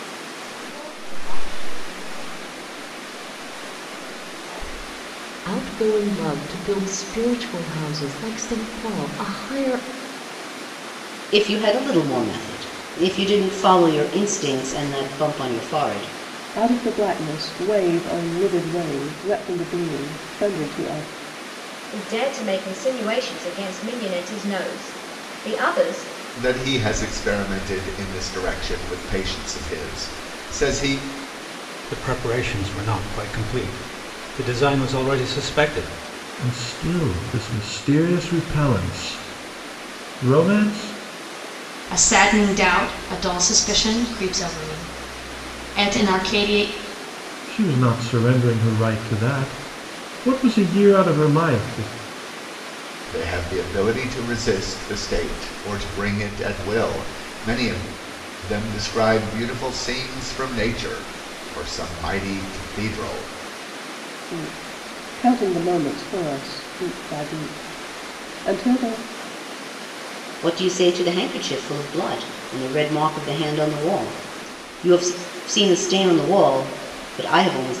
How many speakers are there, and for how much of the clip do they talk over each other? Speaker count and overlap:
nine, no overlap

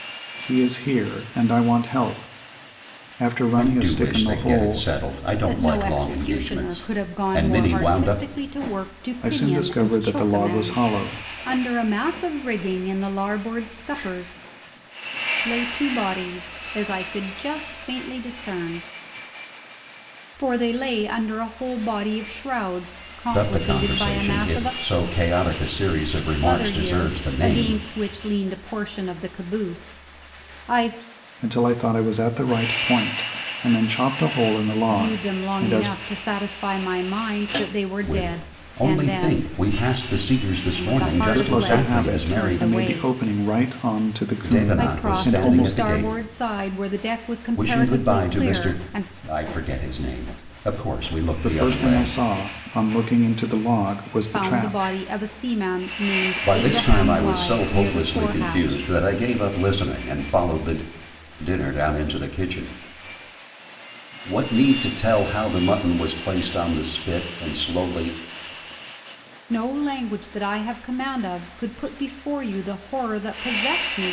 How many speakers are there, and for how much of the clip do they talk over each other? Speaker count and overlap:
three, about 28%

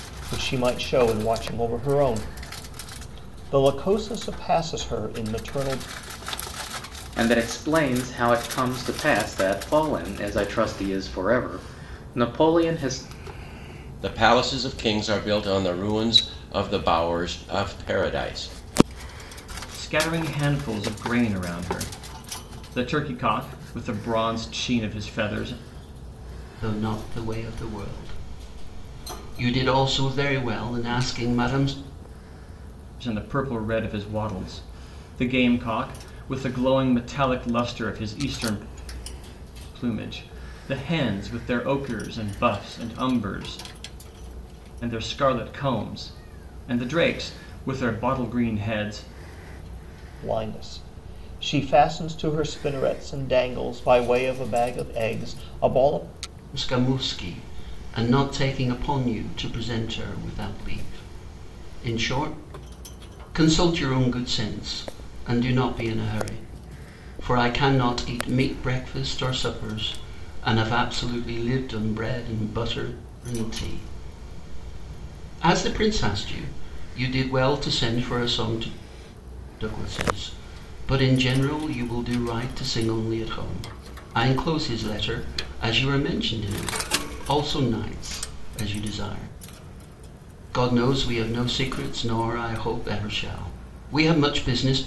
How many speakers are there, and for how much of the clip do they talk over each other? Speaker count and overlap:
five, no overlap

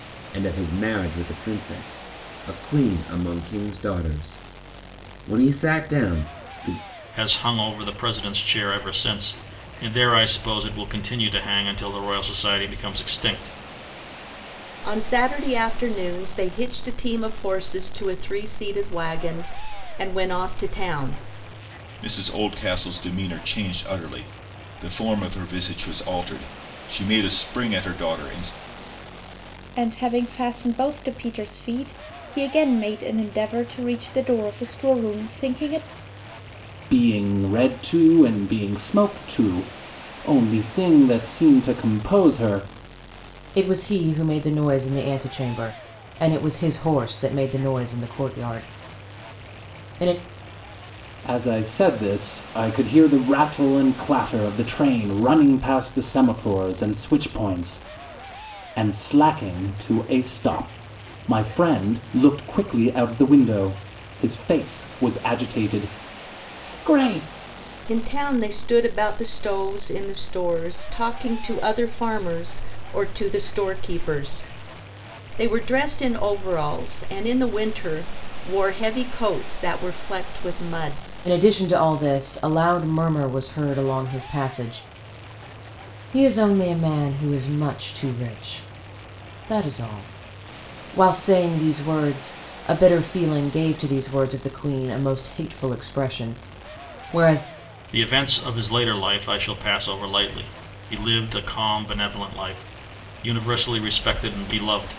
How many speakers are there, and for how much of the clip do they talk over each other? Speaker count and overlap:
seven, no overlap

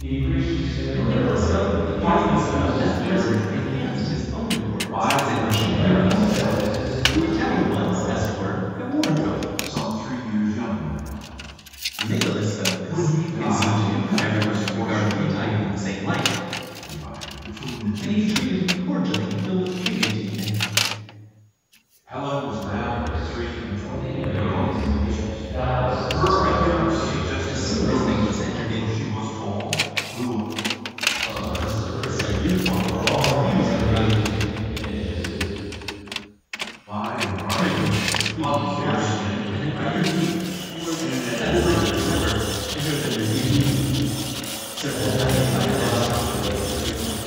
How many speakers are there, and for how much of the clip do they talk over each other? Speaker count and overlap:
three, about 57%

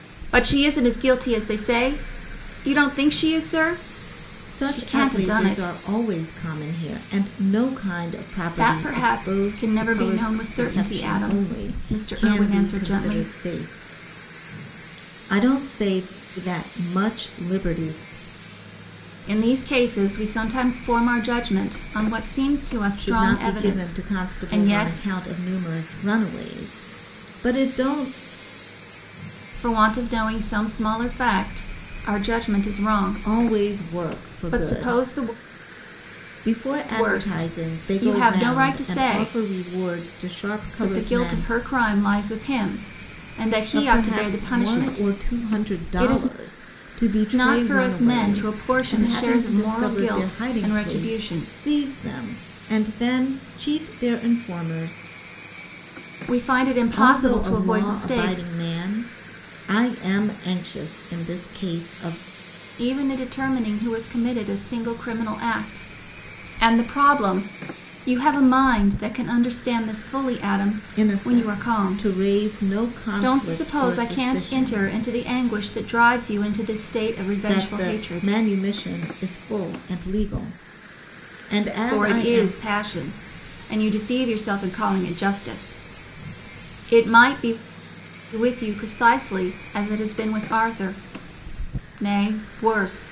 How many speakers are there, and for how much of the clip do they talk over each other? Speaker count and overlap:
two, about 29%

